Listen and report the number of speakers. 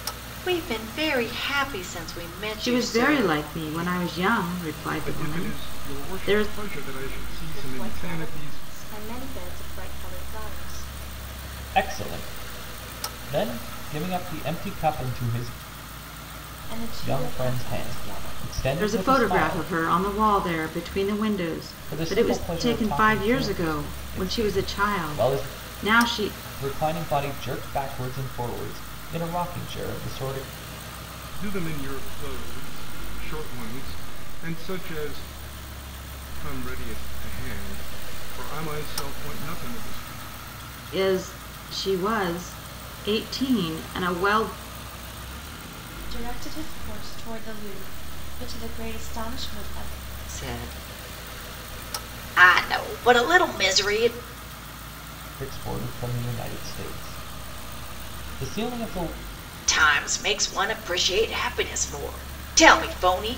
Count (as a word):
six